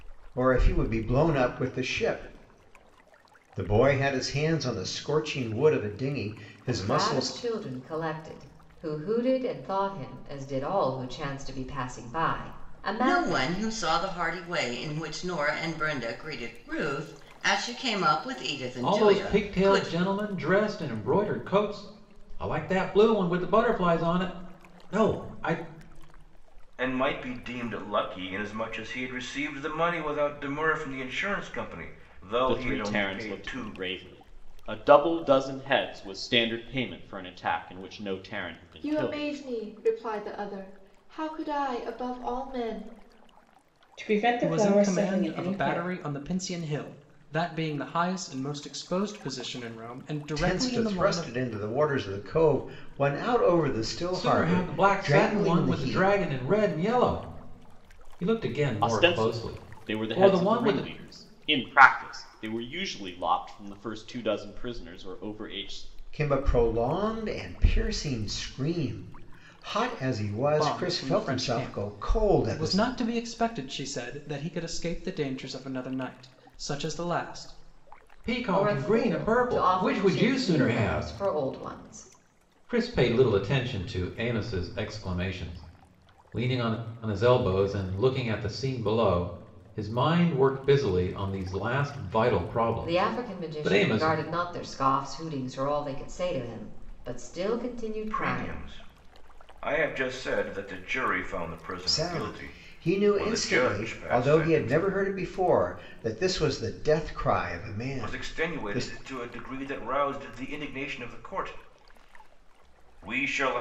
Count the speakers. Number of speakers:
nine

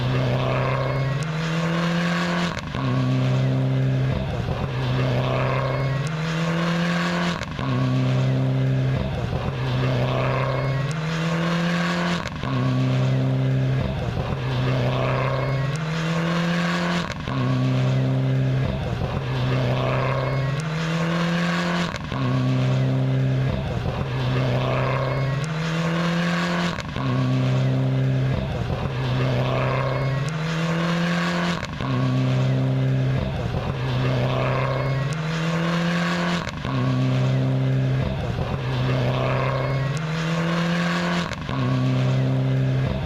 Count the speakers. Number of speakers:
zero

